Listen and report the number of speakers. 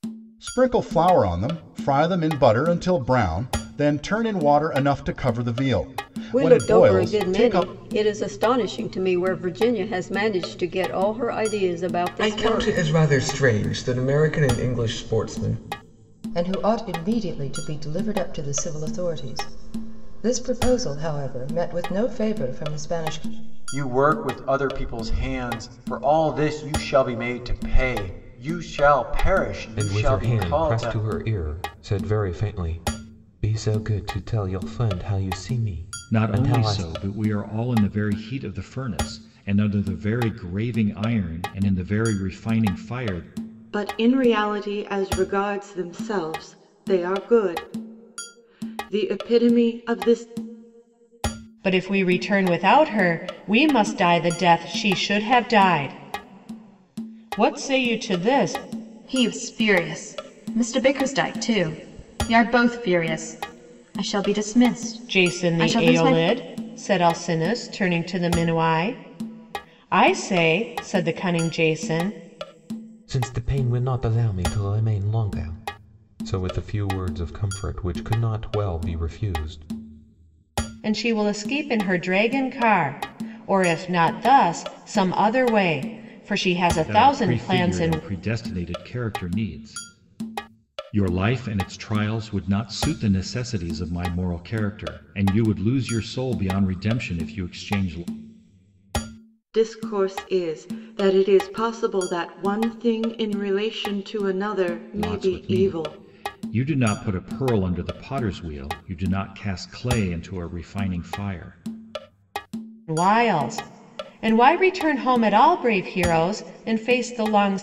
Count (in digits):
10